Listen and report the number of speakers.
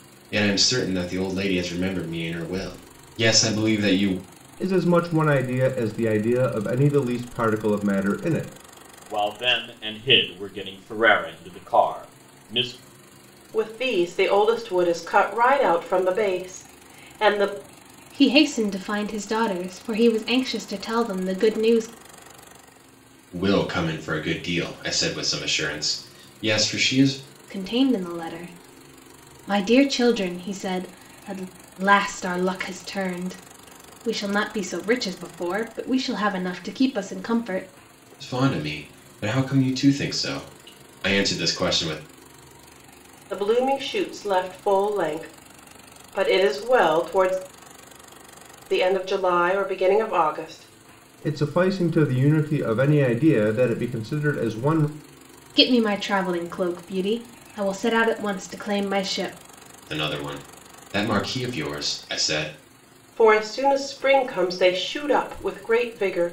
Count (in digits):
5